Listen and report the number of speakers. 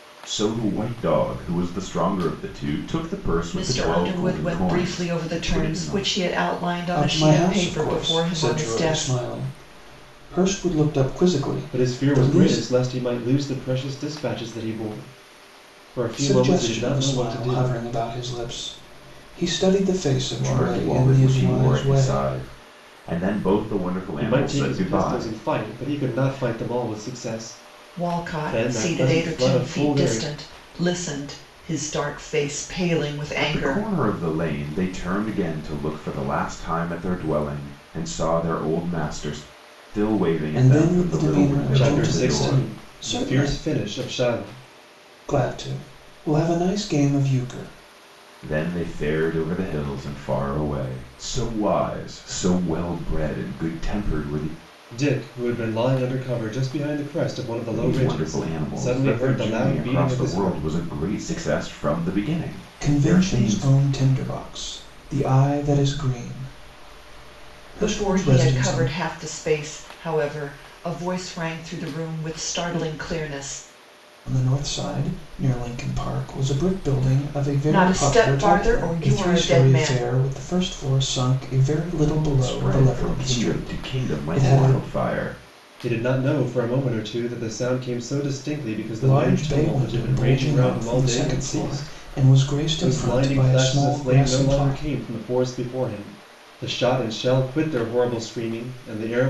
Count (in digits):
4